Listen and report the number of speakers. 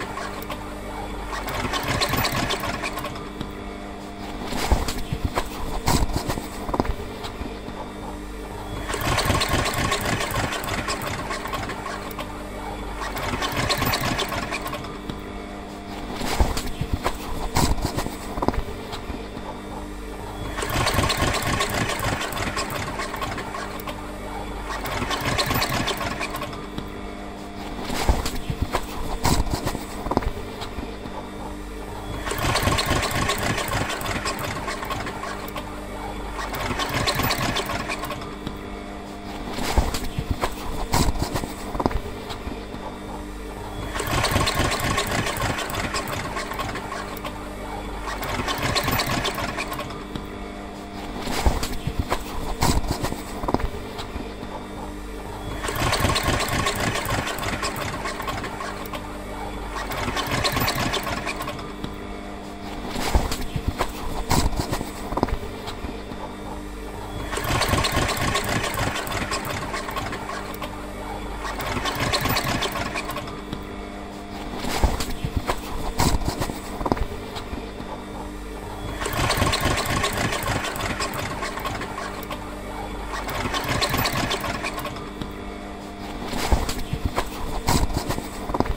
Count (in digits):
0